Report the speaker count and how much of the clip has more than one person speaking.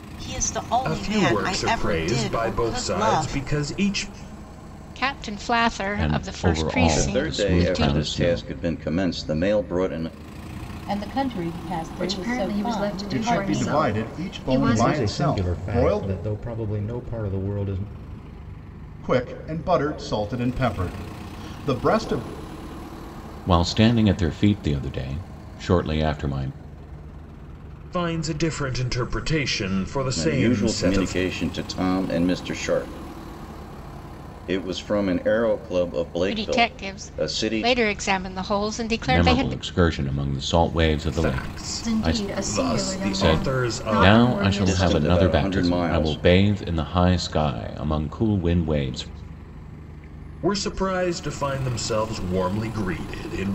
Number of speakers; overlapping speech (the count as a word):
nine, about 32%